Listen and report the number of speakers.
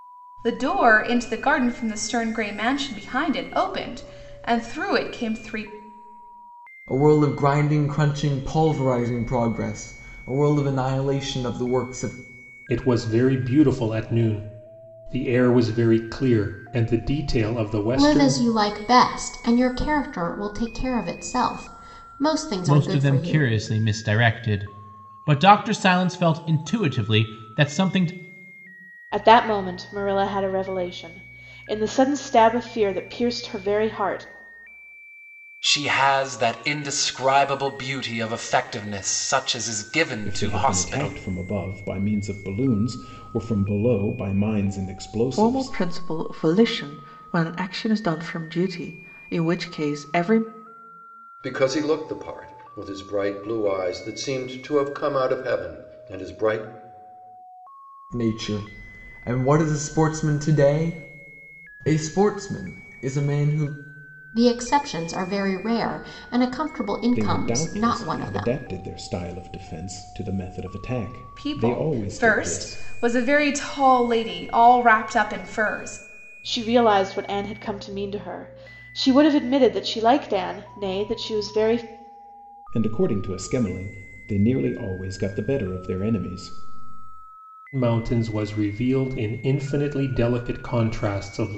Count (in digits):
10